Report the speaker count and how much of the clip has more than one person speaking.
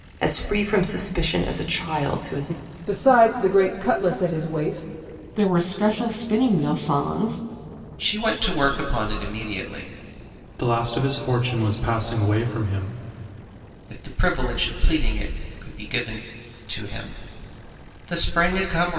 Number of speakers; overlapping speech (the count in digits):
5, no overlap